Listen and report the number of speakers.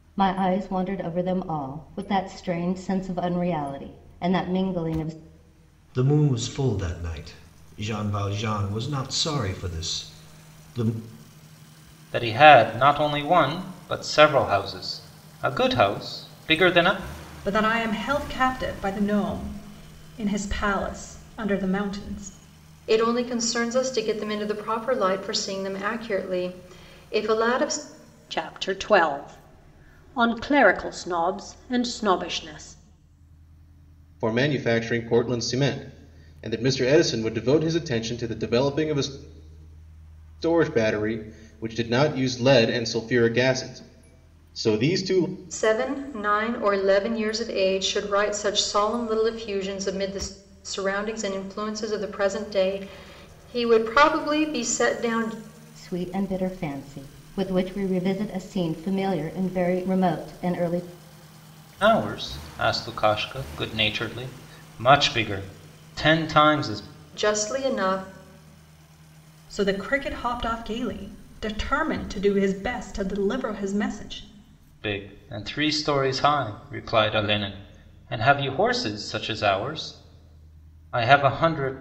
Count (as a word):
seven